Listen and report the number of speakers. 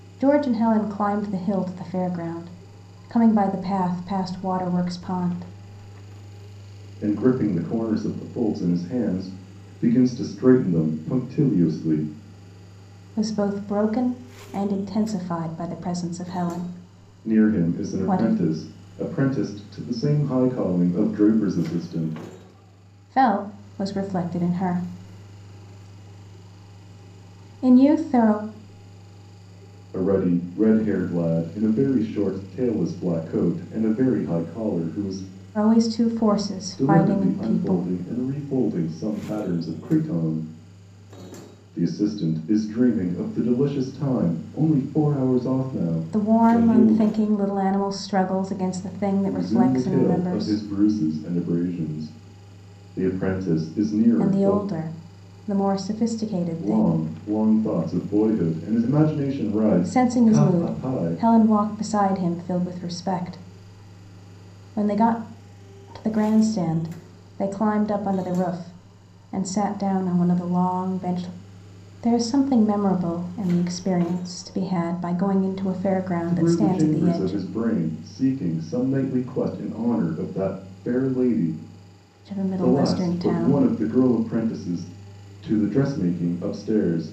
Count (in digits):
2